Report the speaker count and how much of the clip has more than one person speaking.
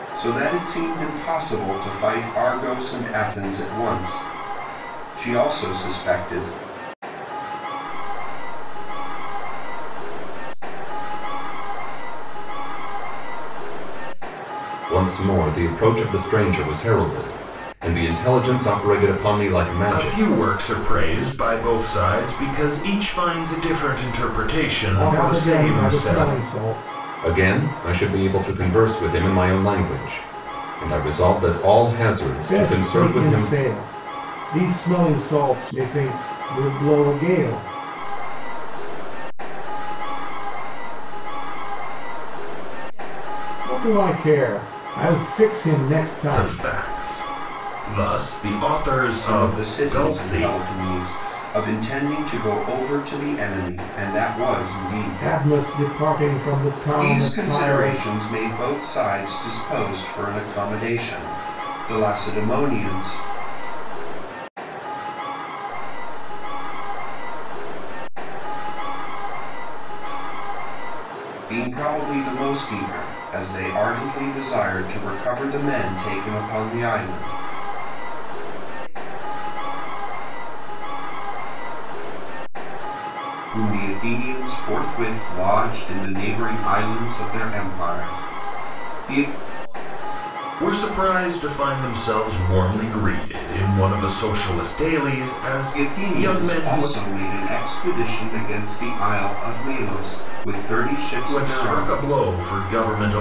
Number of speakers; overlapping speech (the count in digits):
5, about 11%